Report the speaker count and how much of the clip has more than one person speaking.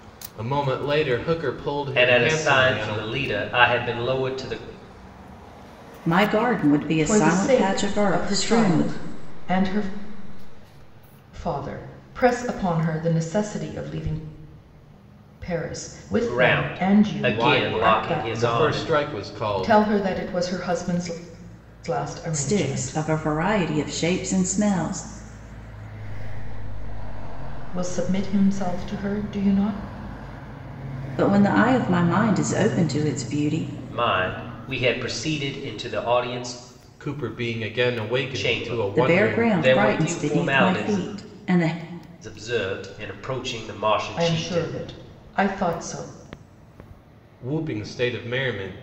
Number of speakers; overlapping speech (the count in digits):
5, about 26%